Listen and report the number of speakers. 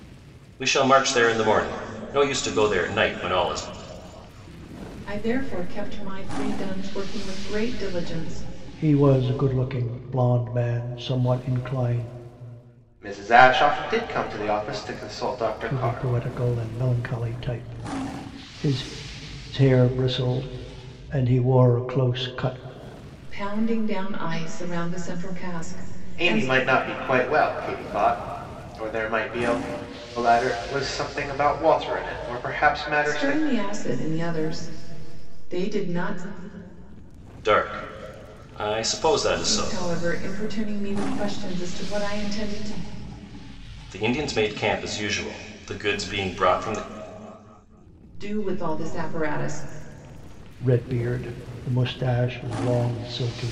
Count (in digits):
4